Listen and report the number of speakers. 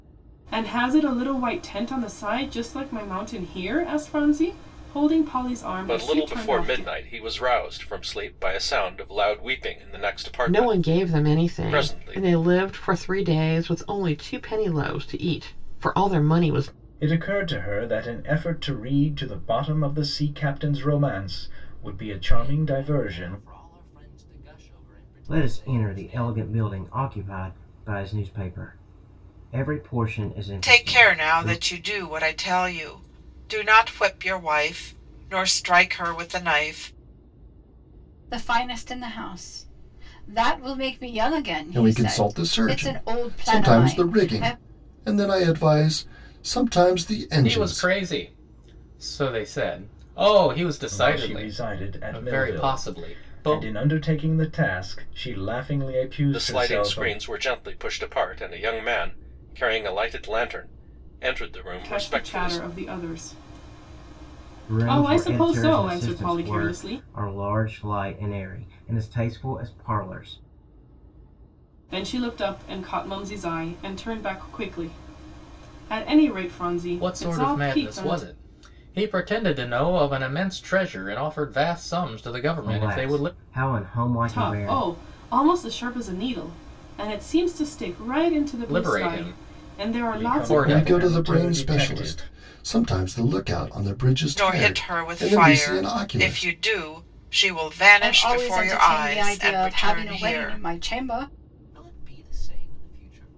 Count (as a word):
ten